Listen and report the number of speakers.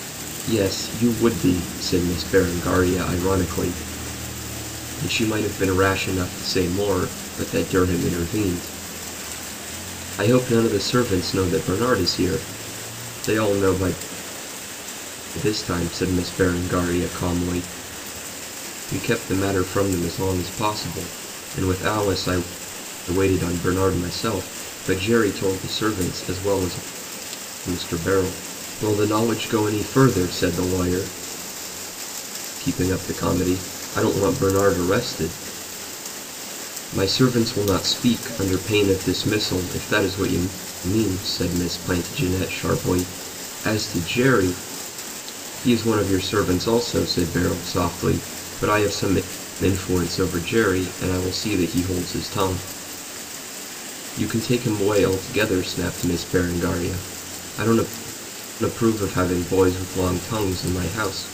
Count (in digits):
1